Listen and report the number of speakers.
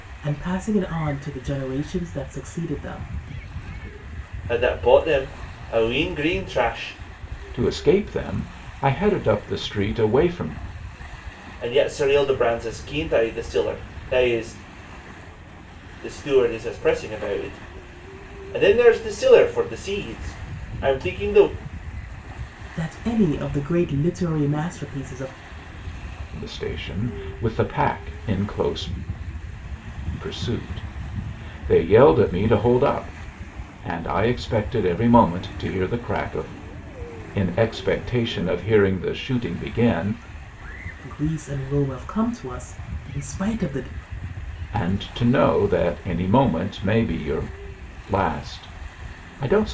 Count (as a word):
three